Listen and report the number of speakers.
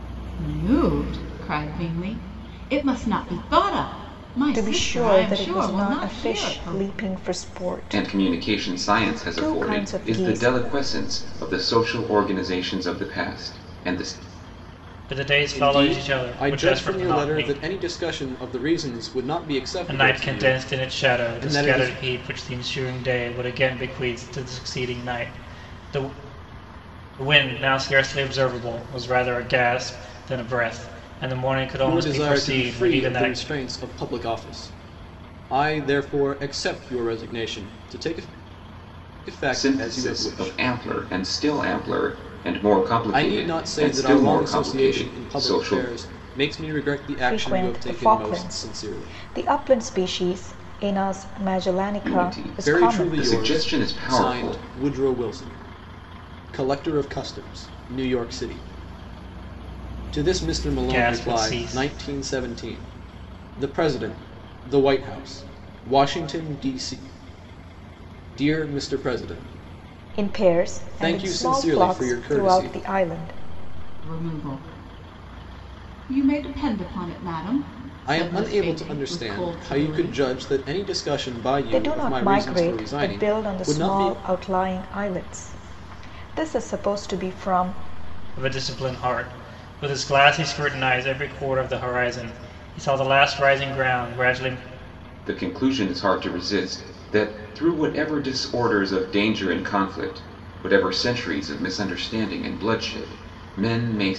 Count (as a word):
five